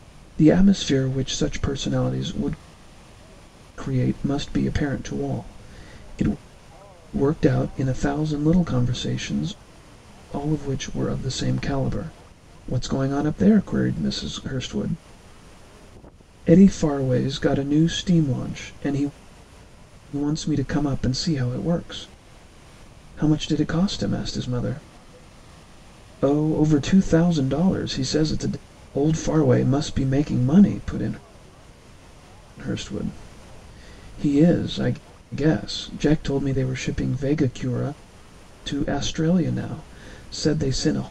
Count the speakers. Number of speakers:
one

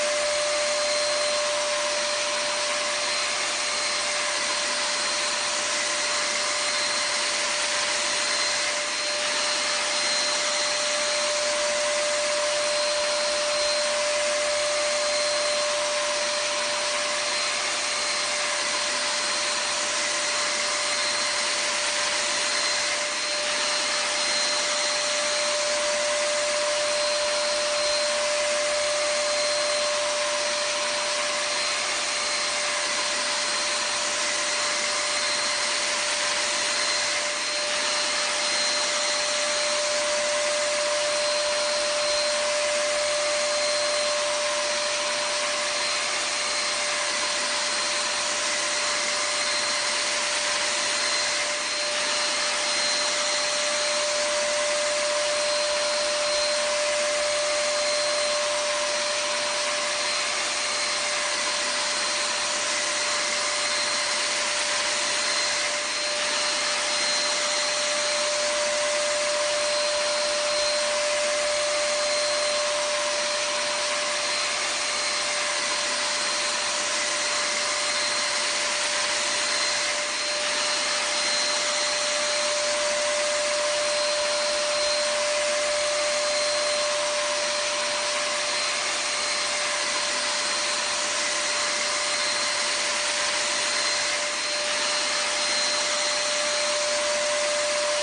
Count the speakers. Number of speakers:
zero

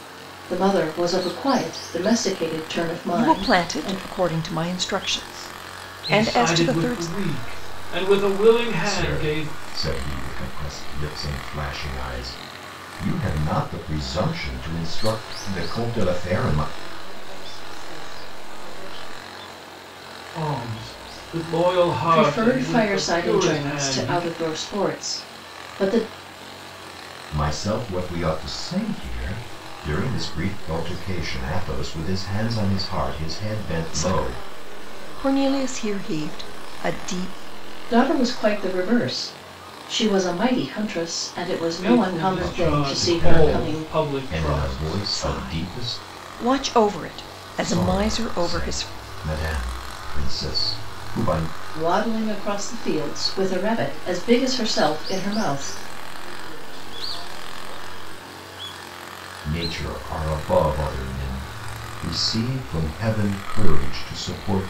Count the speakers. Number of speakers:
five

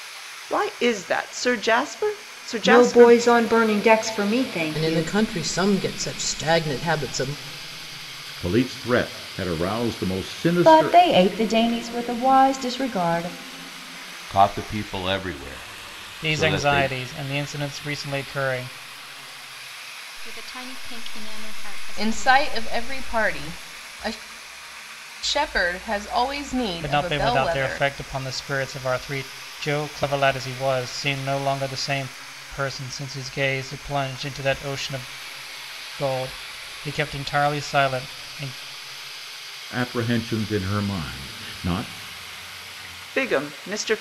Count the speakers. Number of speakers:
nine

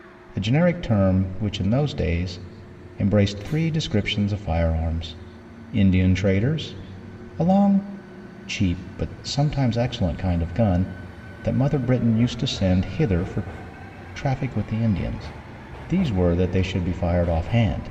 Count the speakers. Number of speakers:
one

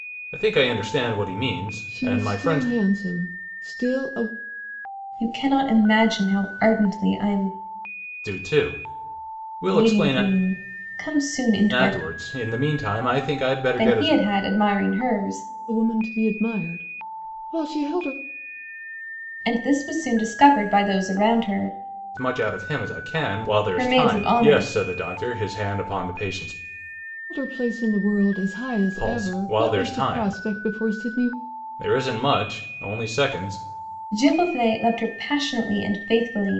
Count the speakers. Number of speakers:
three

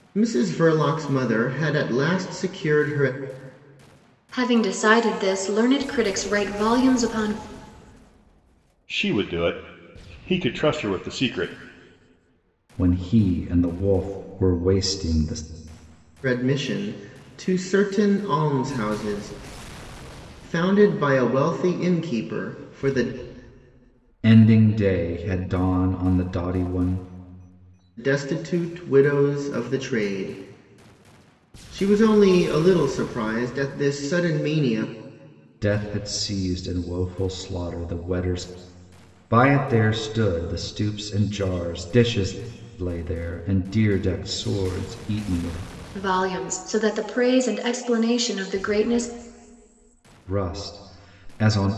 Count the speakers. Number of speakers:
four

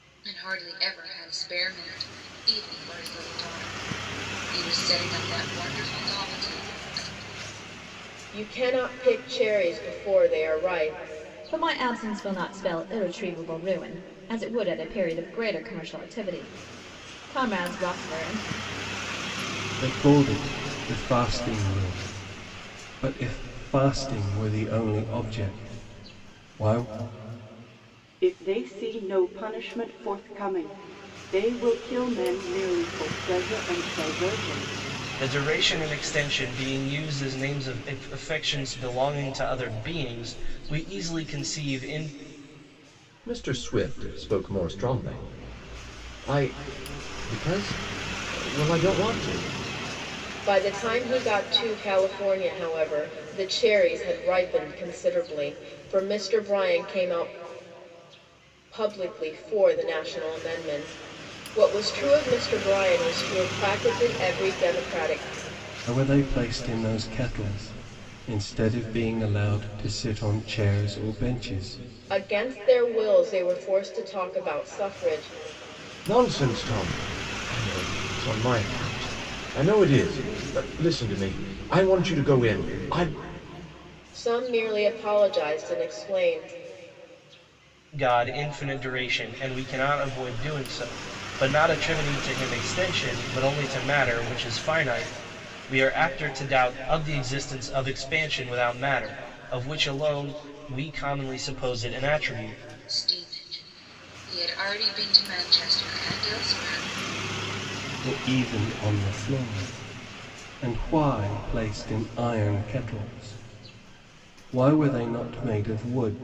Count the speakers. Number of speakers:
seven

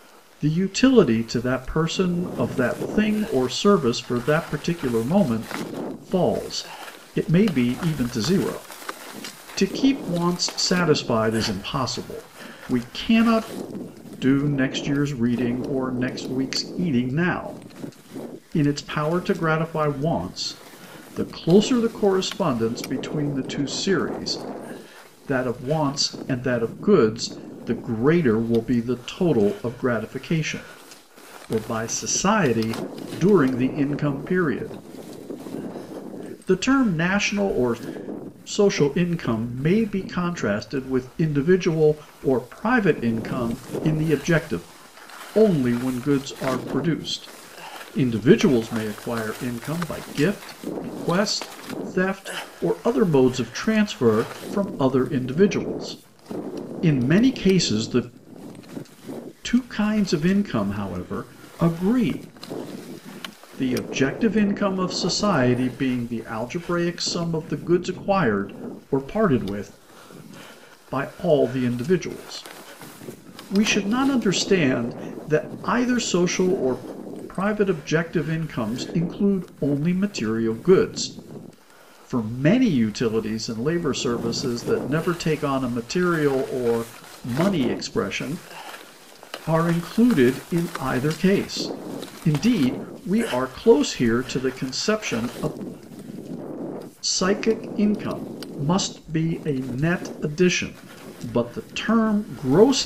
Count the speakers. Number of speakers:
one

